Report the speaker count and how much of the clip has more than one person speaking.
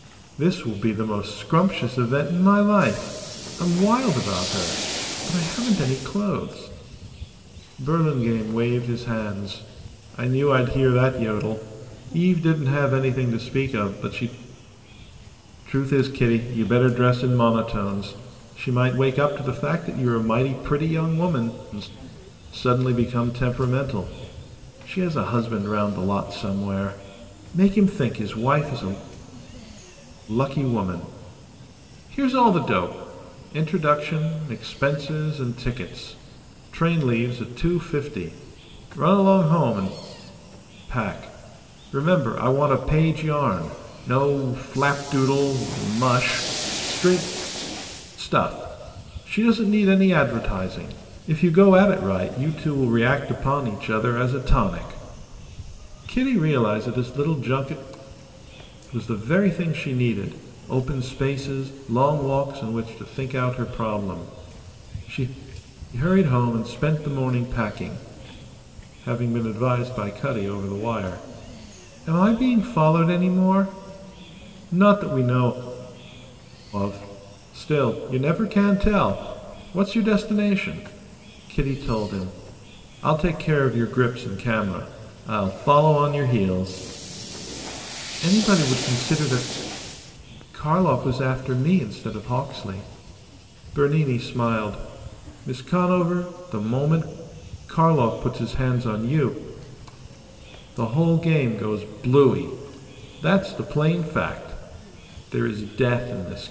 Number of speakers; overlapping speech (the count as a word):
one, no overlap